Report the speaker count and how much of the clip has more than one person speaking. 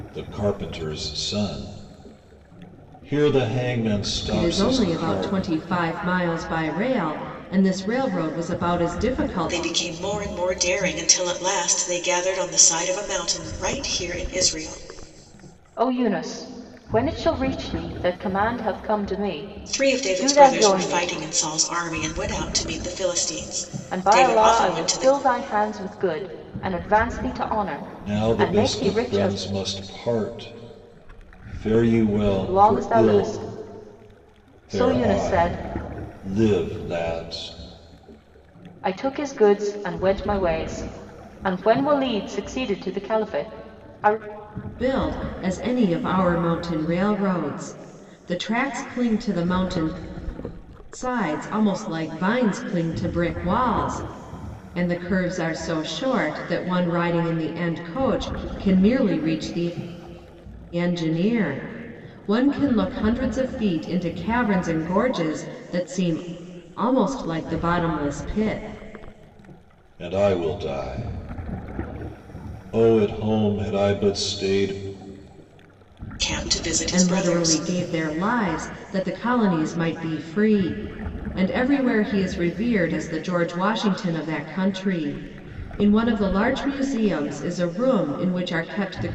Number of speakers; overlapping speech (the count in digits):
4, about 9%